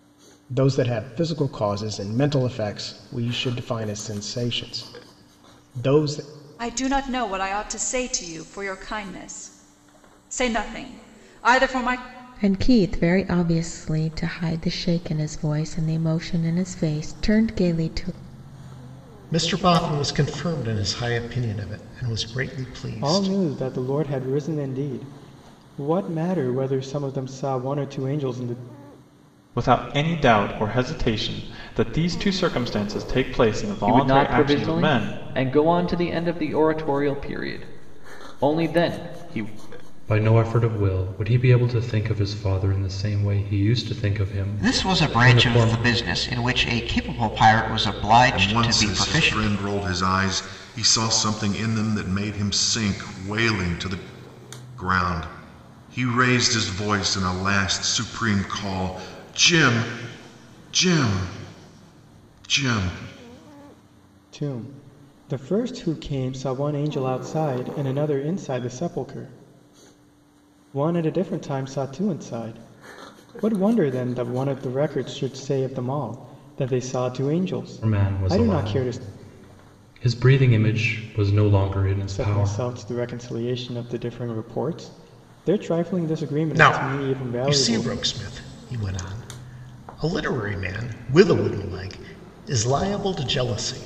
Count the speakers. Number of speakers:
ten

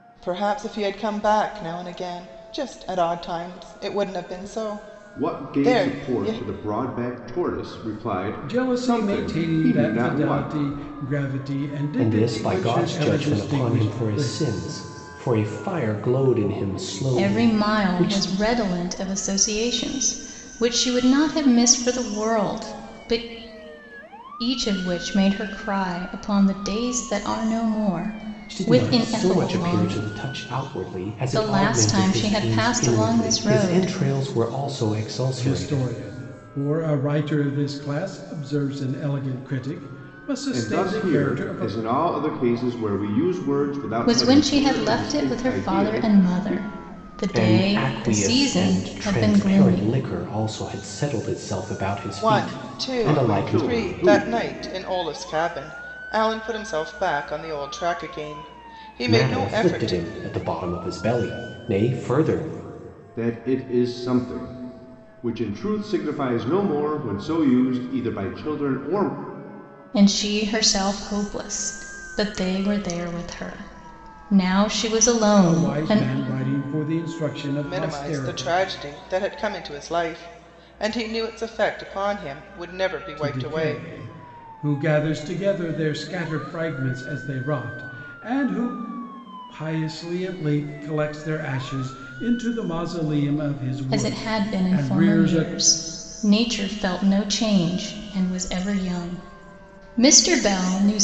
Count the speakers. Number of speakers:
five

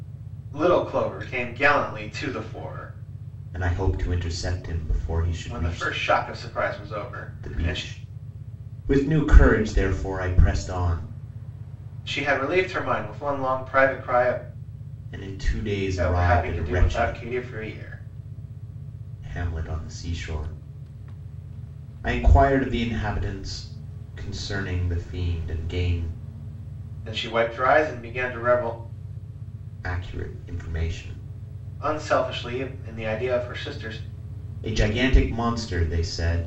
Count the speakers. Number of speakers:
two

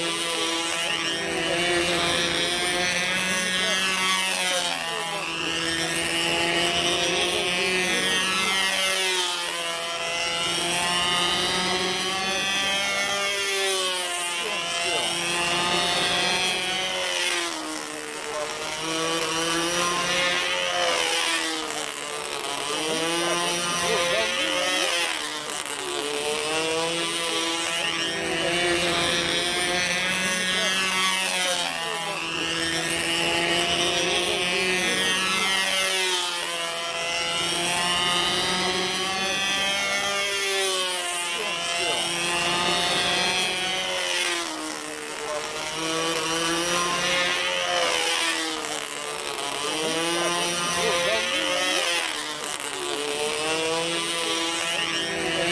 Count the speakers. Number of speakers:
zero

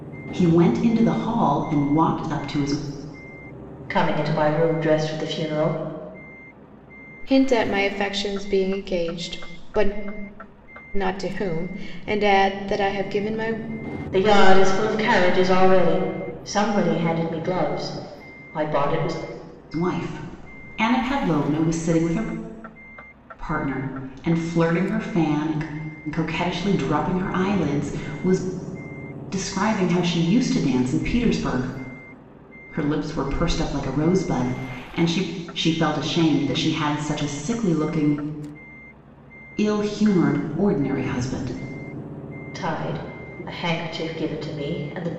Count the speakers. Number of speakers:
three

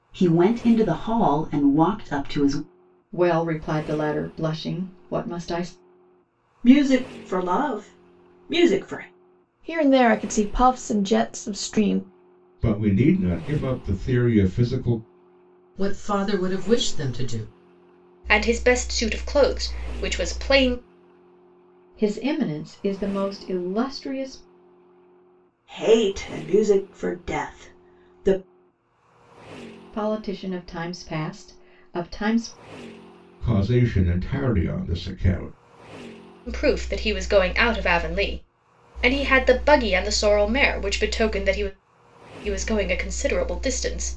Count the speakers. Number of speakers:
seven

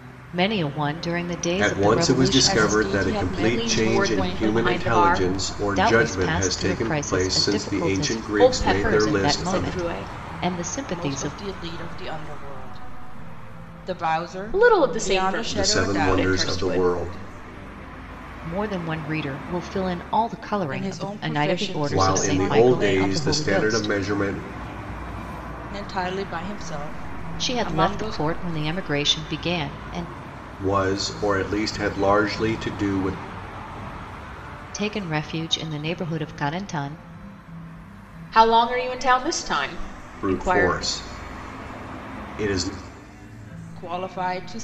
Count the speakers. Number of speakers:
four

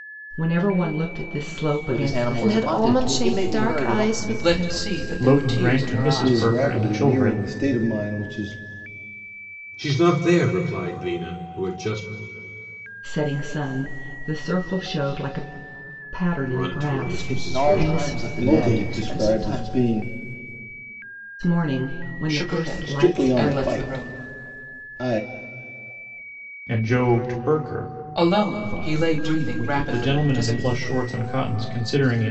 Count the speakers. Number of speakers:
eight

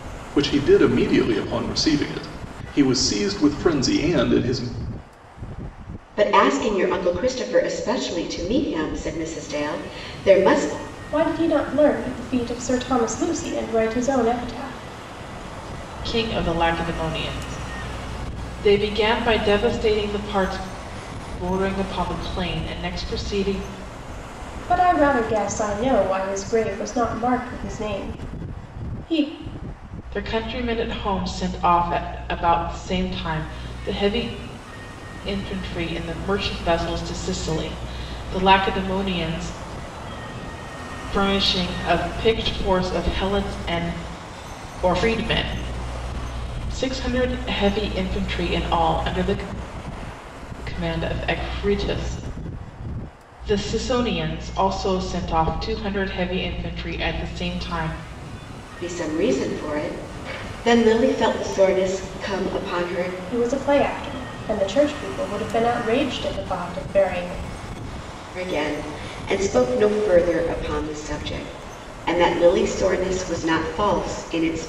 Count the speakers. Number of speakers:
four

